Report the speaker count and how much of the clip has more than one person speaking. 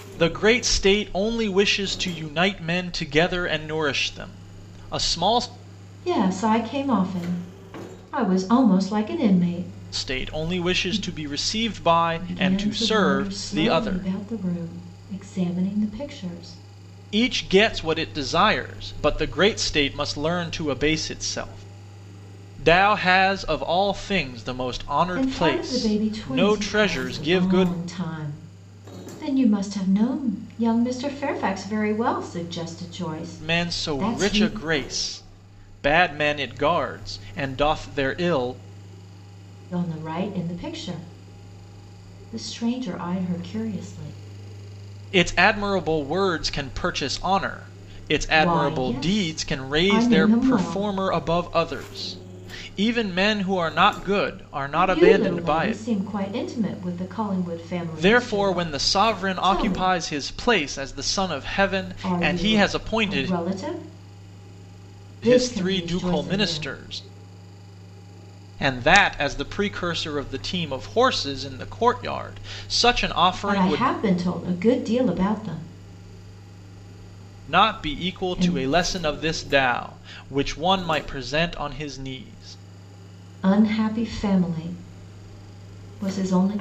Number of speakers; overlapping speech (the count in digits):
2, about 19%